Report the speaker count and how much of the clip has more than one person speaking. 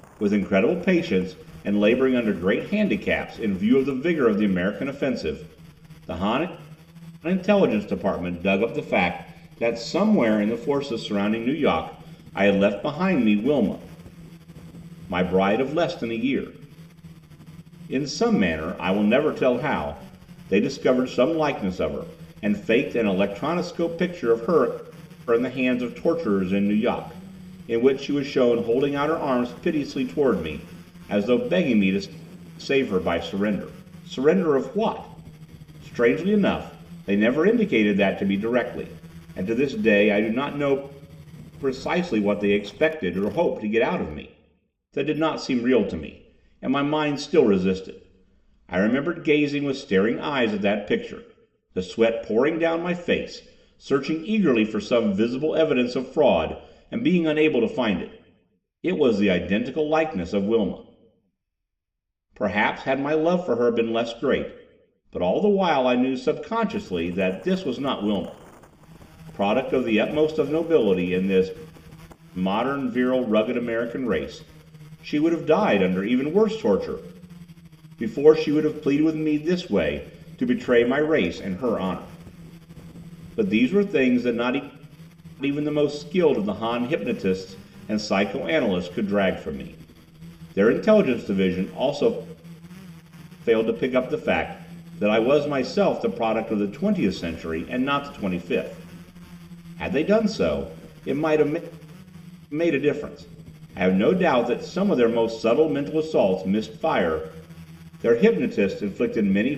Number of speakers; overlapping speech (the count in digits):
1, no overlap